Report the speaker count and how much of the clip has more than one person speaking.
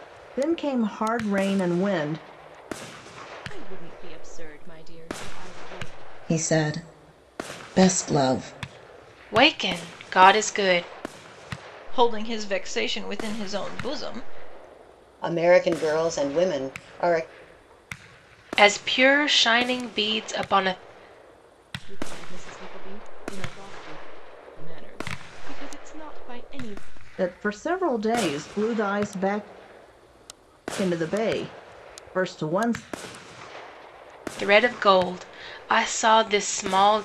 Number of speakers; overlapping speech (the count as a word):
six, no overlap